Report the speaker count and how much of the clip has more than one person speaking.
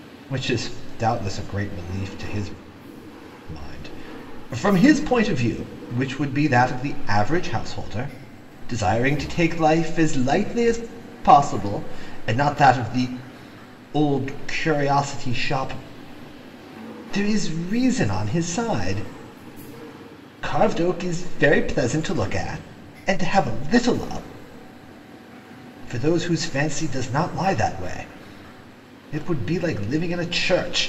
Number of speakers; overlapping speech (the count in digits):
1, no overlap